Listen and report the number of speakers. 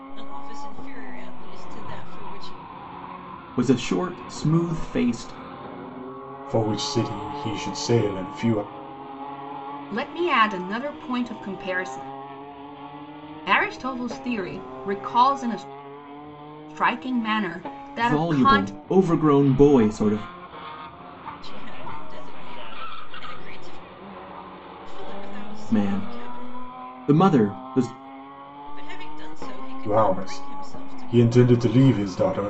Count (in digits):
4